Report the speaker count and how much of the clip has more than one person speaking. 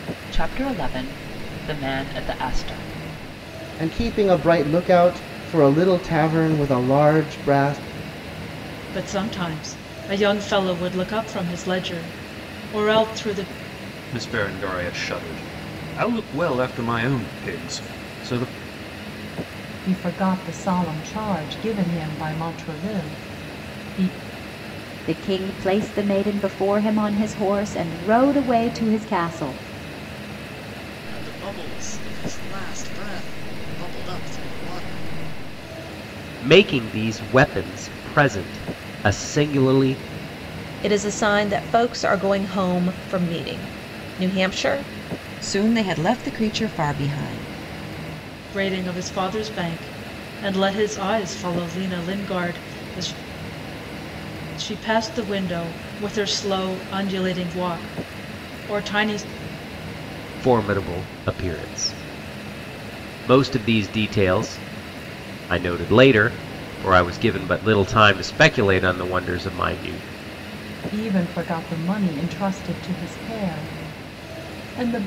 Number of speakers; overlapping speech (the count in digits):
10, no overlap